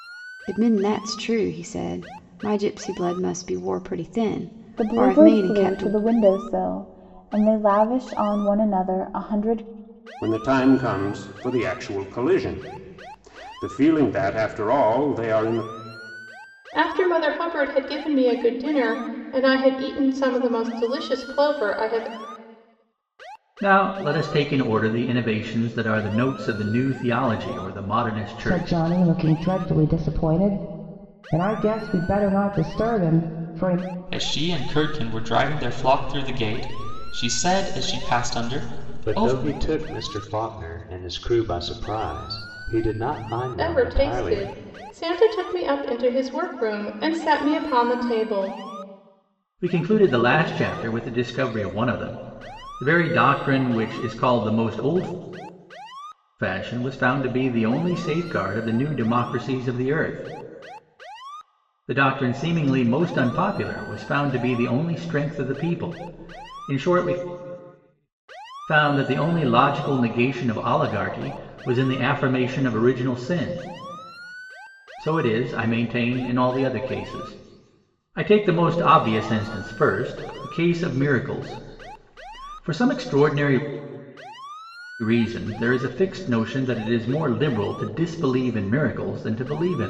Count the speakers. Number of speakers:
8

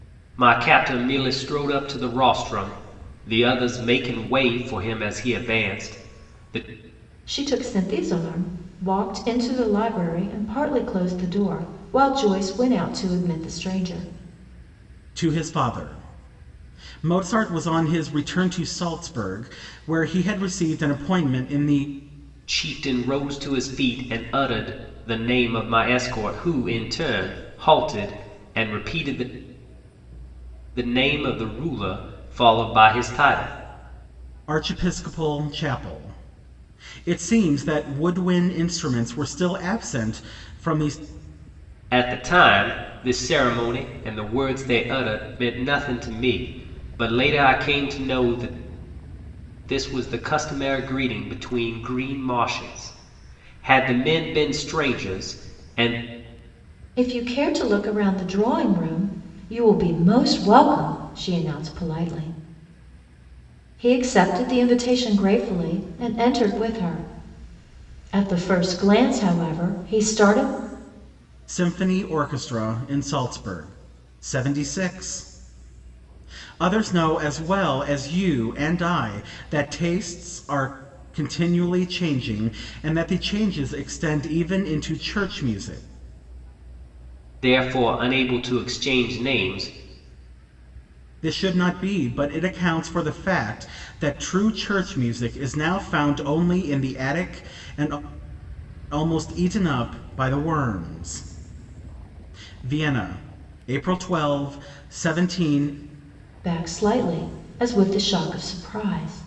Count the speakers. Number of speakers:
3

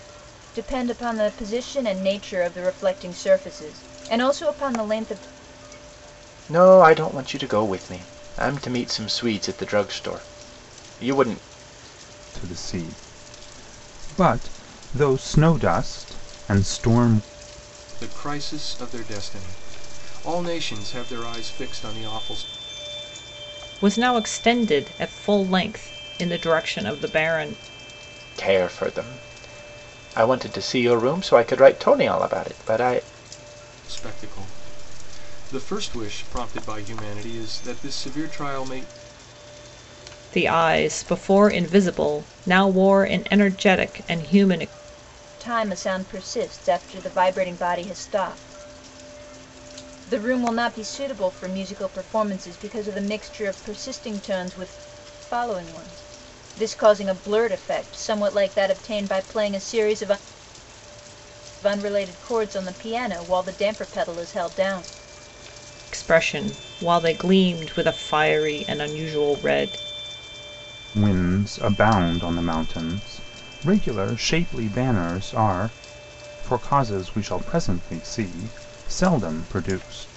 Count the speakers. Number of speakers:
5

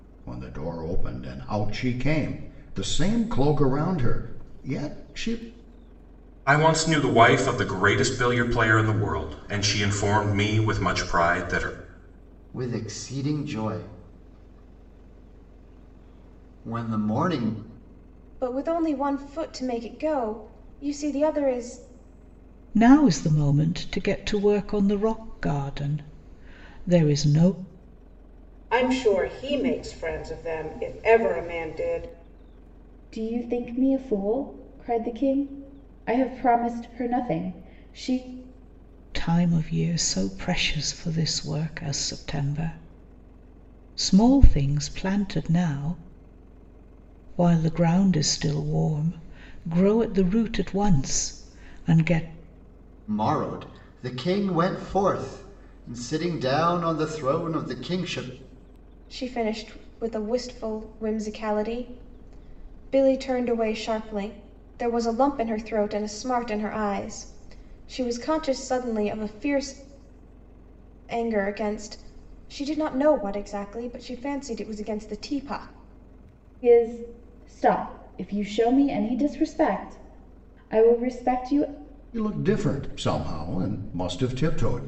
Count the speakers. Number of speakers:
7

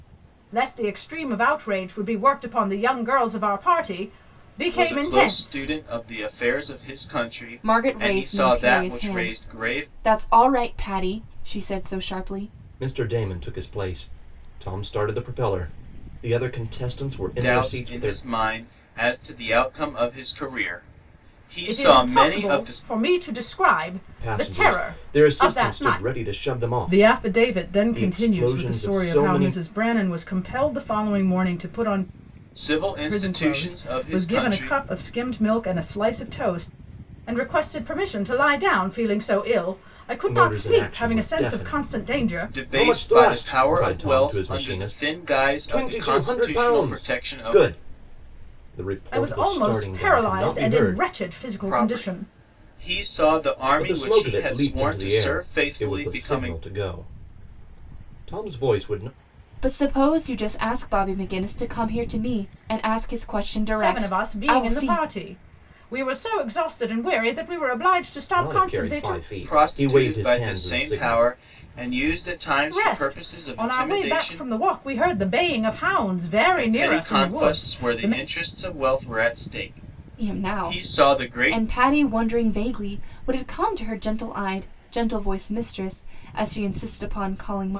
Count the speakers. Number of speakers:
4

